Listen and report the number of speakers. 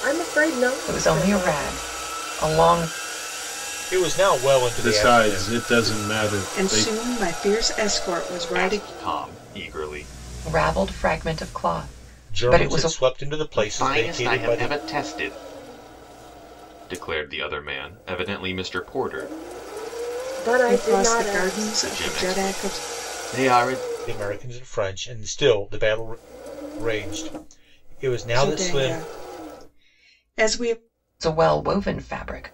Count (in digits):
6